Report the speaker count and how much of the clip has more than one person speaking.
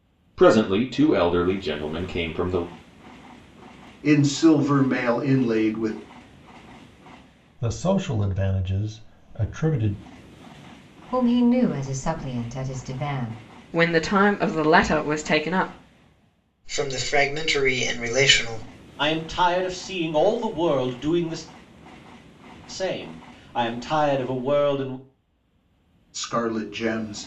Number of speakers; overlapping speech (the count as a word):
seven, no overlap